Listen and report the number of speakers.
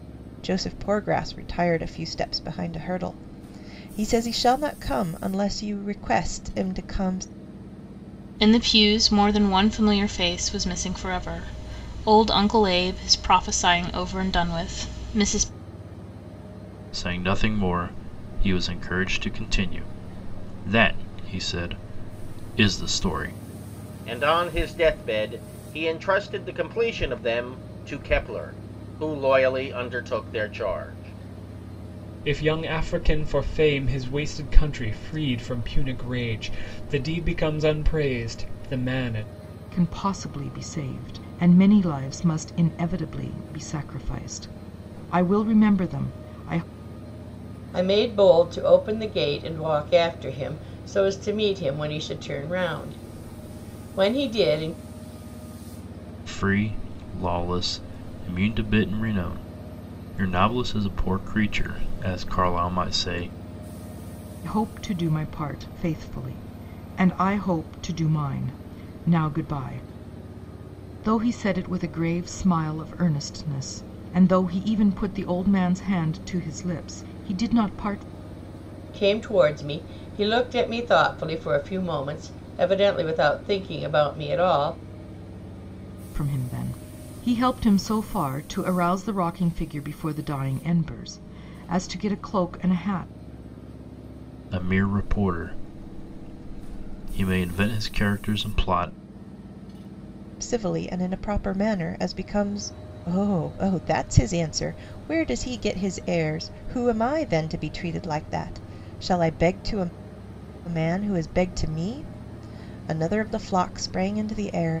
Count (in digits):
7